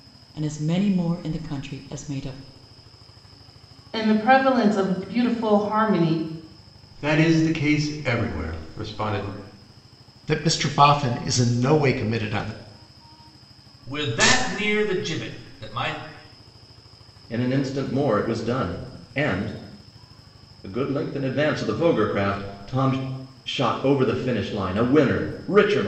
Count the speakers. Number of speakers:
six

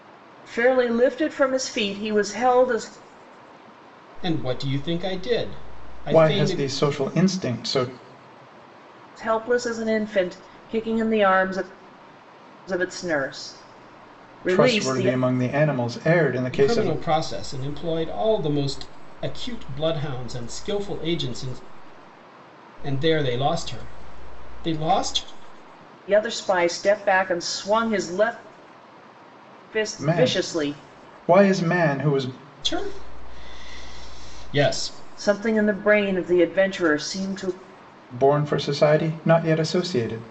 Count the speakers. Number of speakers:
three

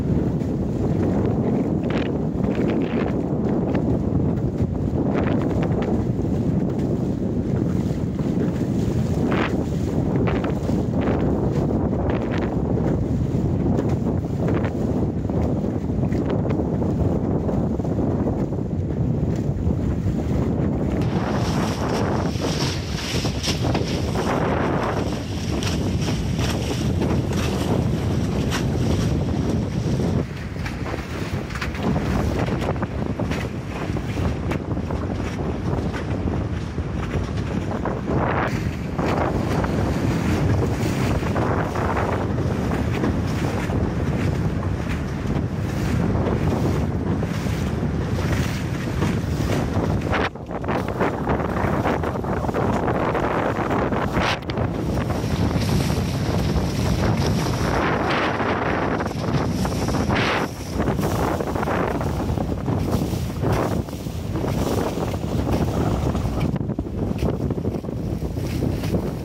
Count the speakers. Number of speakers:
zero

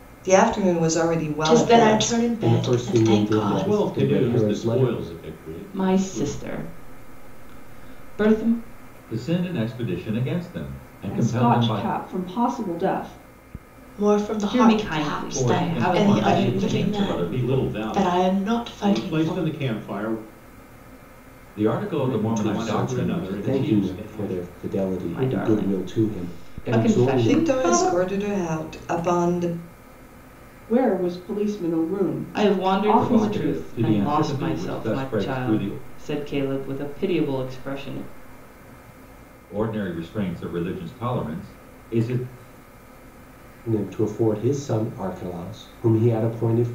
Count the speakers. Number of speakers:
seven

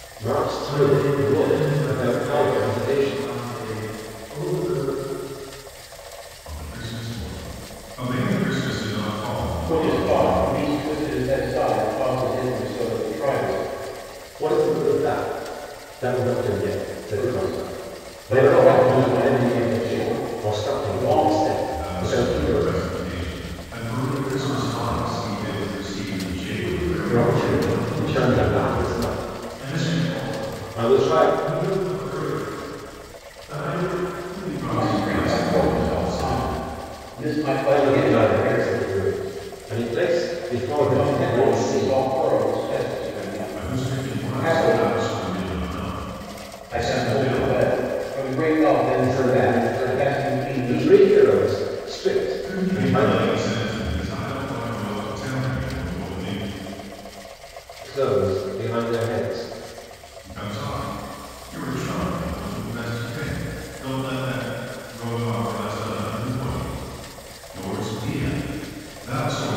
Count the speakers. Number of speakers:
four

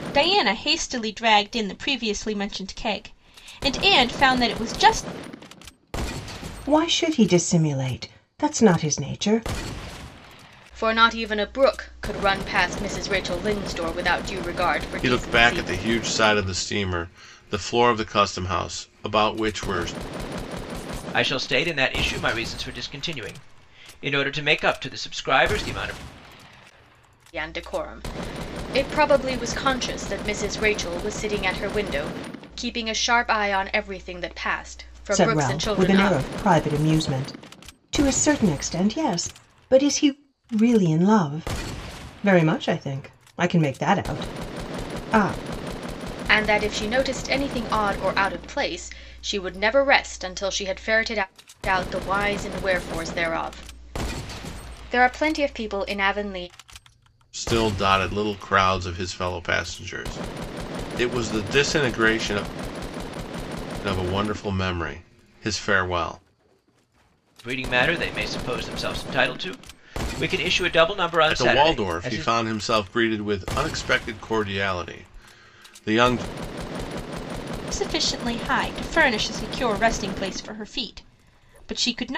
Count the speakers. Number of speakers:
five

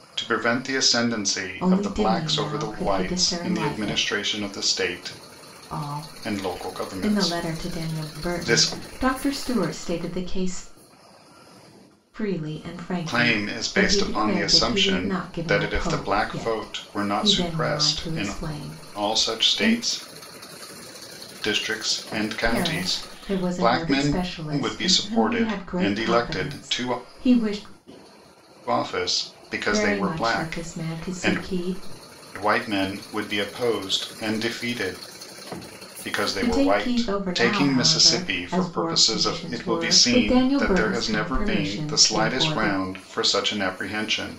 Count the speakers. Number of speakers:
two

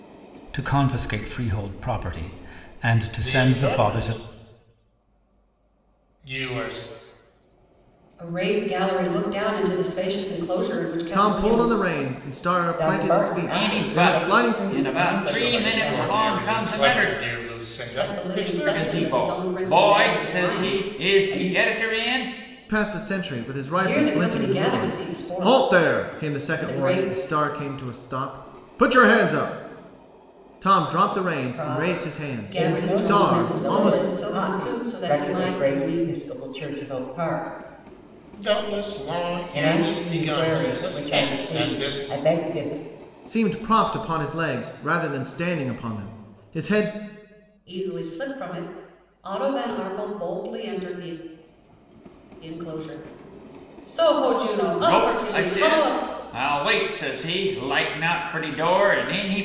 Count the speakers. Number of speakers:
six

